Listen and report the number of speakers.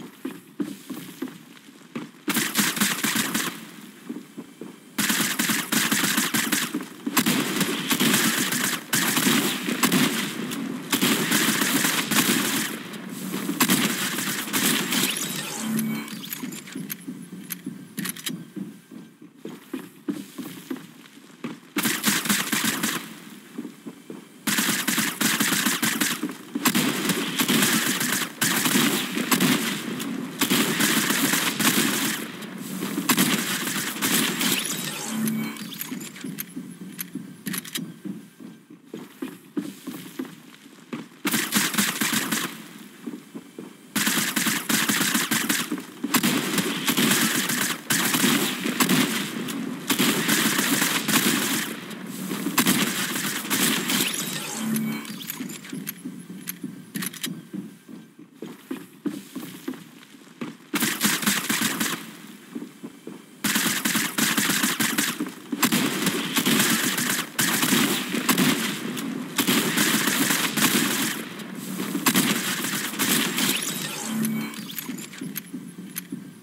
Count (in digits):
0